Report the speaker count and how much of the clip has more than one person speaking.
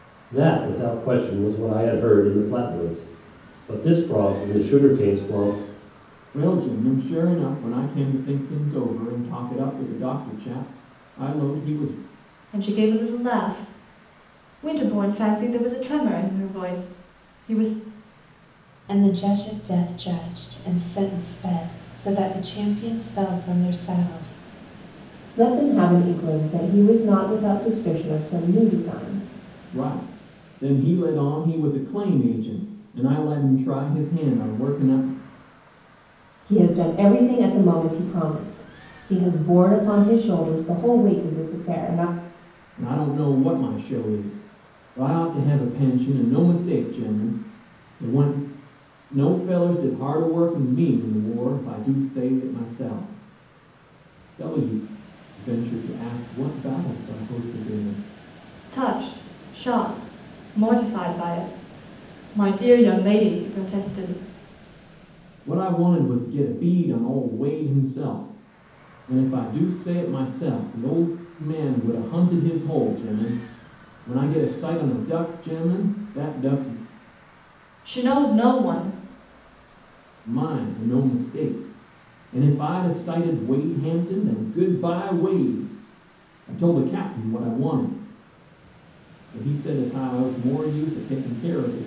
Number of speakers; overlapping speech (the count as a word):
five, no overlap